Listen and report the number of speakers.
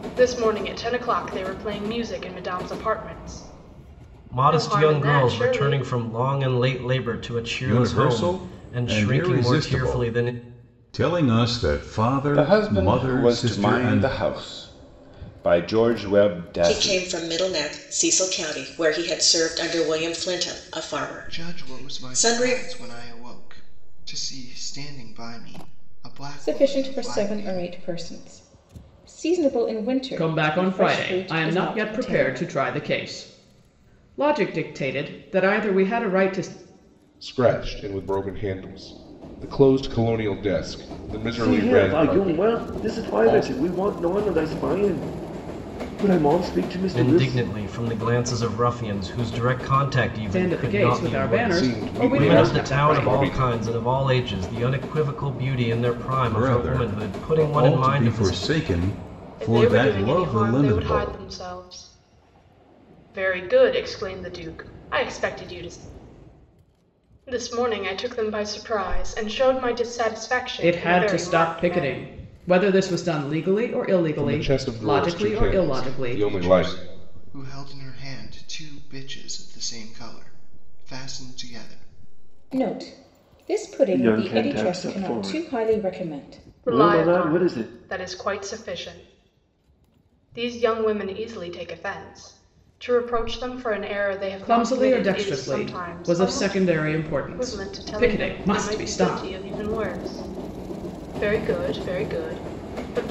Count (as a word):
ten